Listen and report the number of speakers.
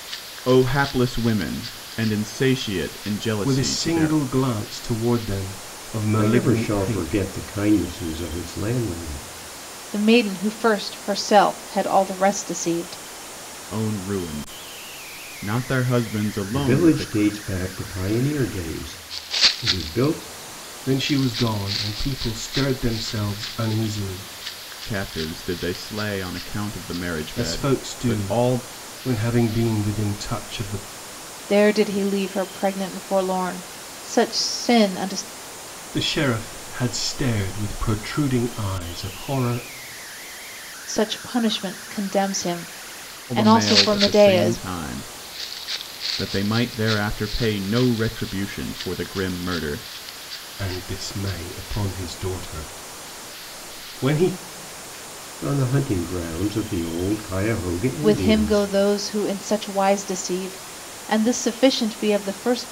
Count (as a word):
four